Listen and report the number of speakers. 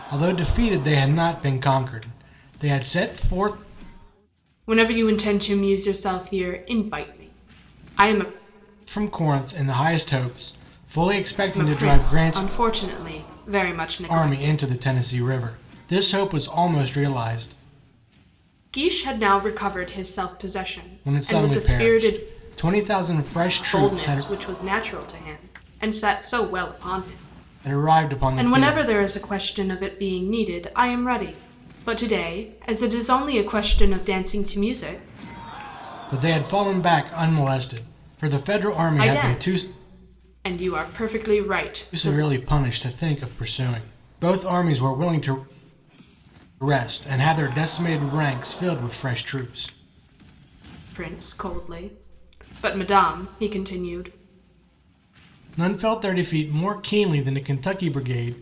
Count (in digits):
2